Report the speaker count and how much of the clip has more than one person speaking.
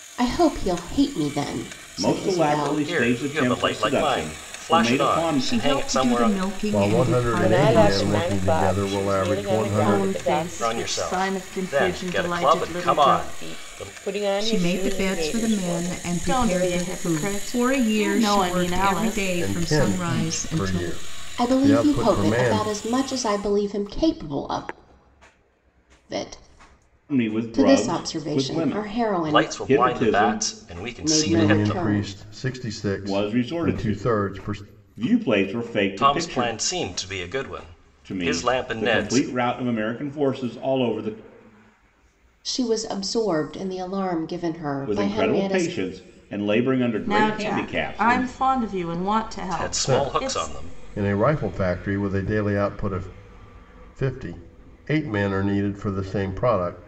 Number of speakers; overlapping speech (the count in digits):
7, about 54%